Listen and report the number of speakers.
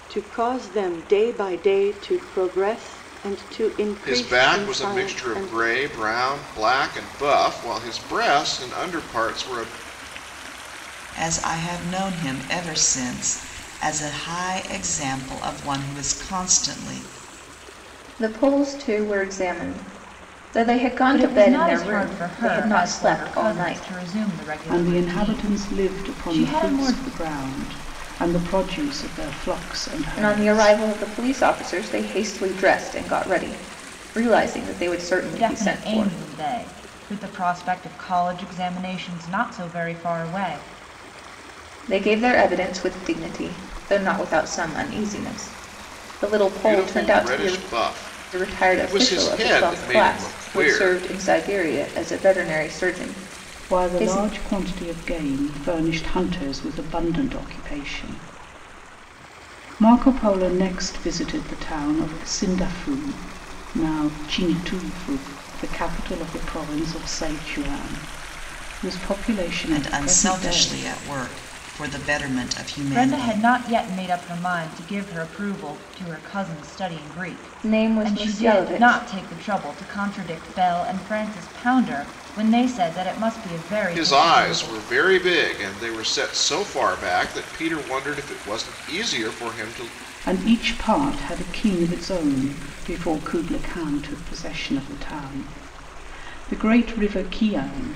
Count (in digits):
6